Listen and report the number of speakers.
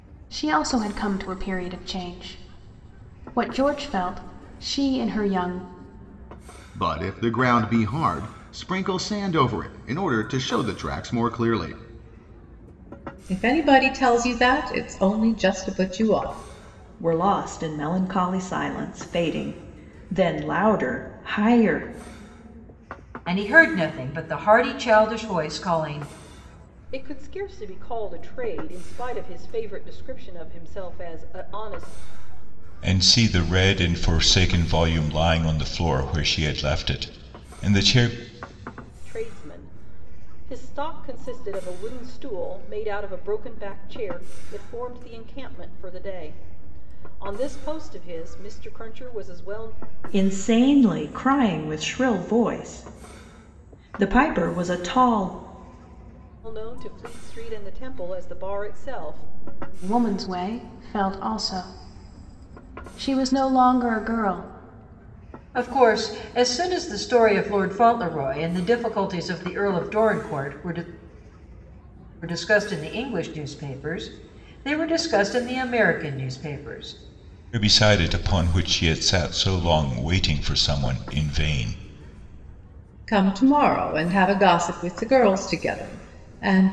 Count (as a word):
seven